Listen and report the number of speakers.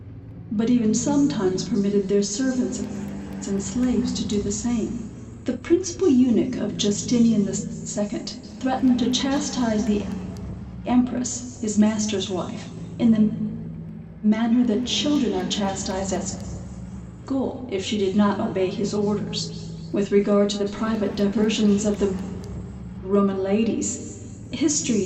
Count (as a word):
one